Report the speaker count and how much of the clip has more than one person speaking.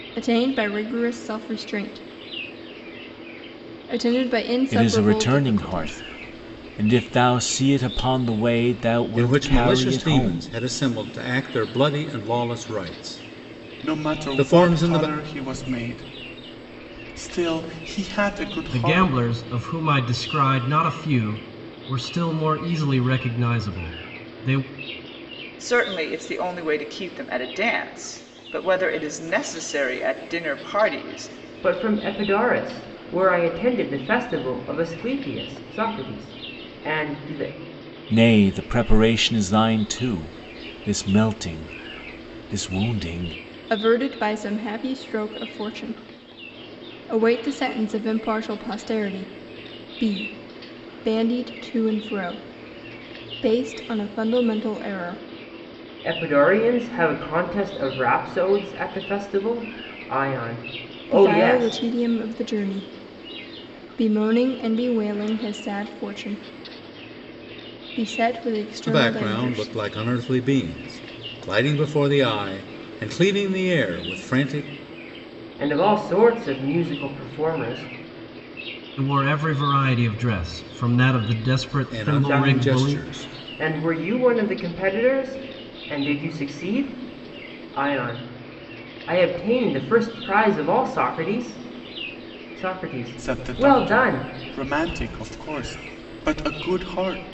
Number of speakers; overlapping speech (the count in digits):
7, about 9%